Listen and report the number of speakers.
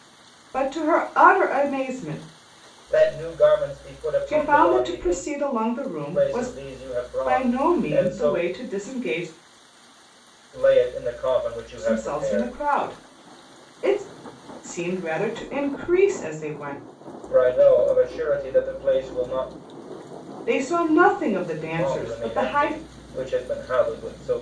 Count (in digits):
2